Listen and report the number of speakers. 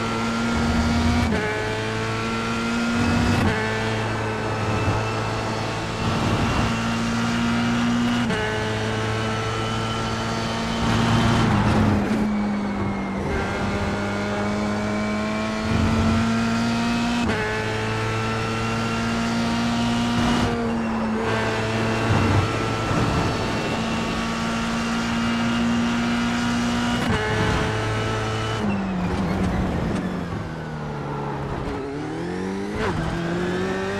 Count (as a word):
zero